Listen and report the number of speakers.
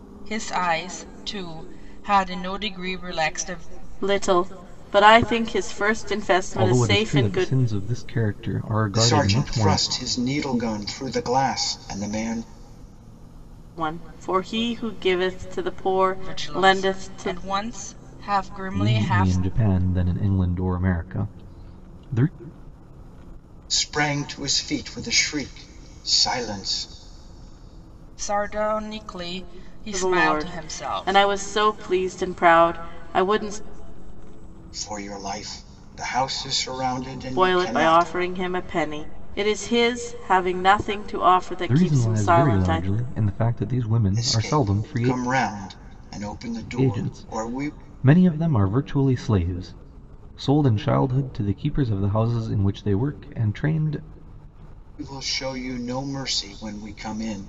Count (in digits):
4